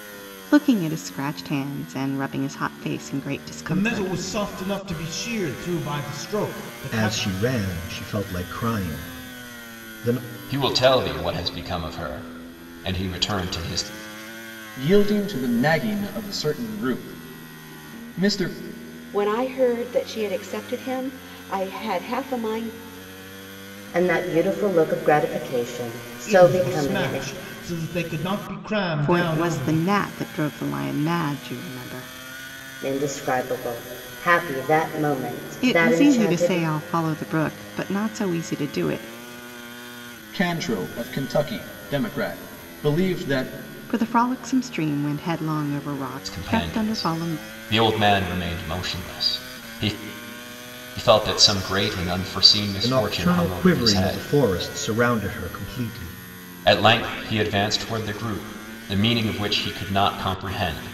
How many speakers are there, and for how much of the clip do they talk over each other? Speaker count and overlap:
7, about 11%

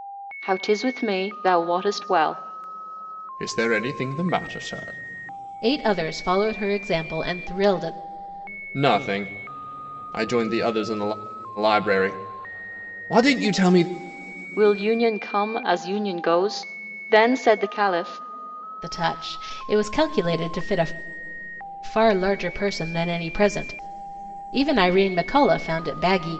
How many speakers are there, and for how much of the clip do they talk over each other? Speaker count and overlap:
3, no overlap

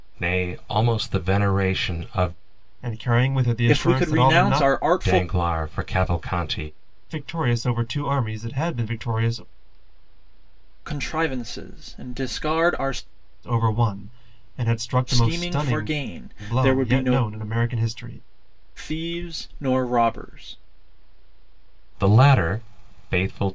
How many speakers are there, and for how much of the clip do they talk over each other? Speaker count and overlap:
3, about 13%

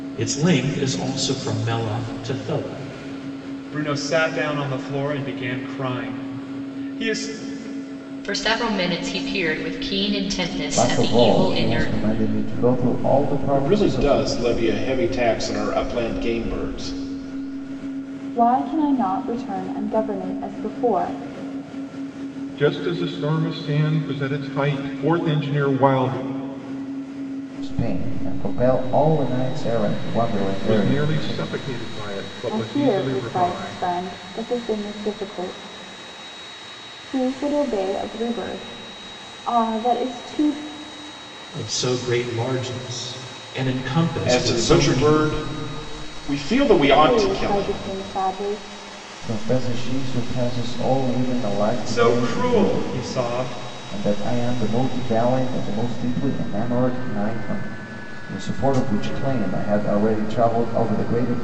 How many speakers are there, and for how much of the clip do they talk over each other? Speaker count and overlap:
7, about 11%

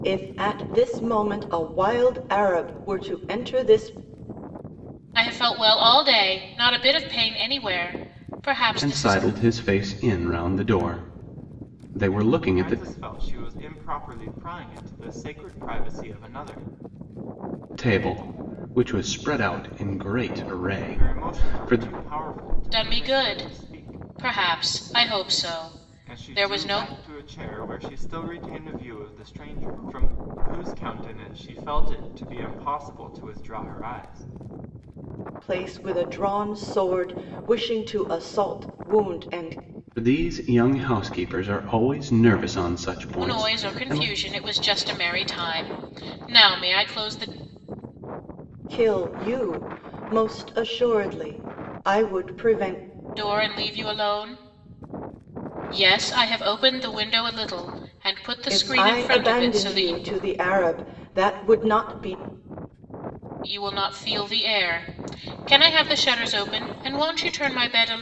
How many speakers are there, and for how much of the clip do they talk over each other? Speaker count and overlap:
4, about 10%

